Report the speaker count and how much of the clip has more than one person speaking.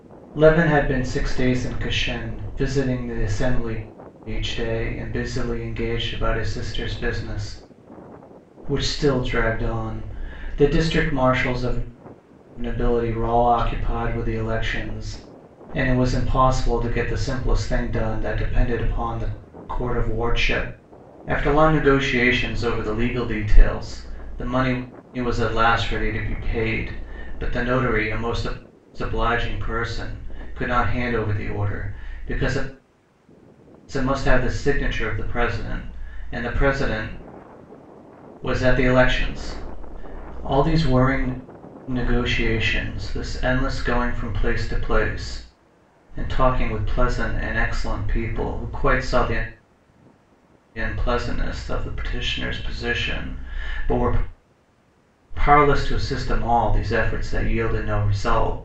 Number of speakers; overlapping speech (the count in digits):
1, no overlap